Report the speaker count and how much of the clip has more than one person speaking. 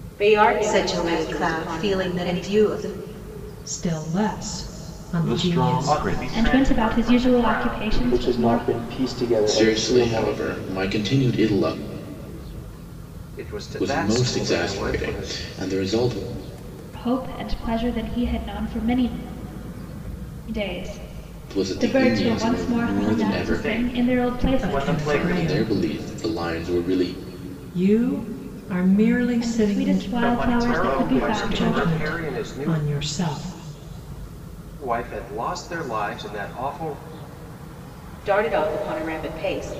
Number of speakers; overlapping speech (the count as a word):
nine, about 39%